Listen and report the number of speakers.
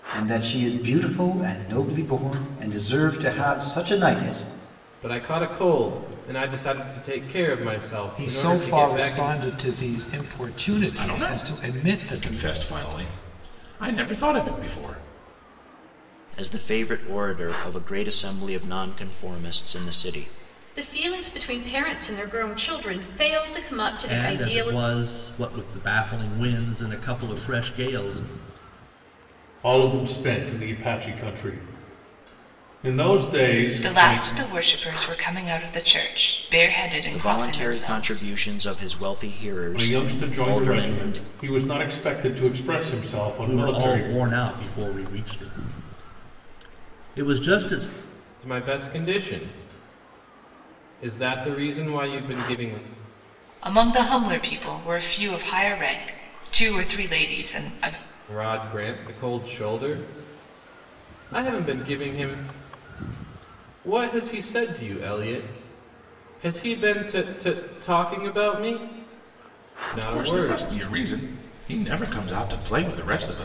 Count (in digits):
9